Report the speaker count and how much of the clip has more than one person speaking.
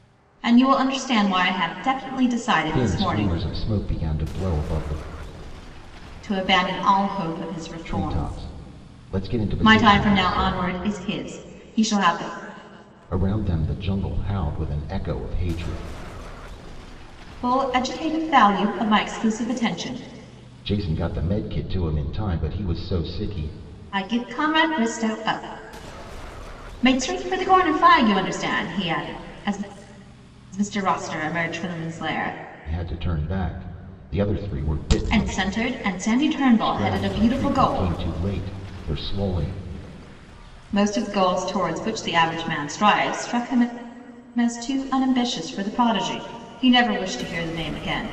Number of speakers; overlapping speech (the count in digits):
2, about 8%